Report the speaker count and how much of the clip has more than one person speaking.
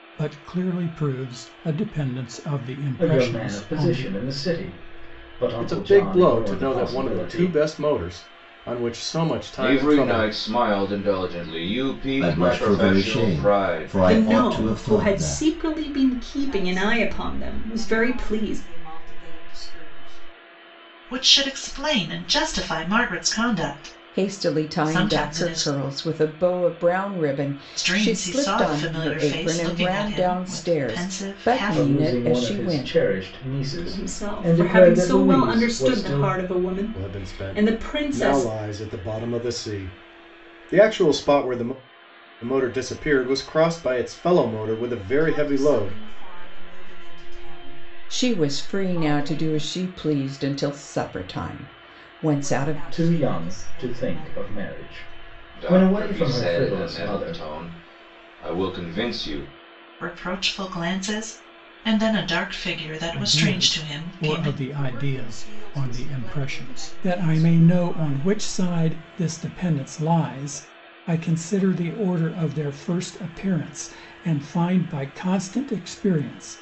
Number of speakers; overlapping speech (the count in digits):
9, about 43%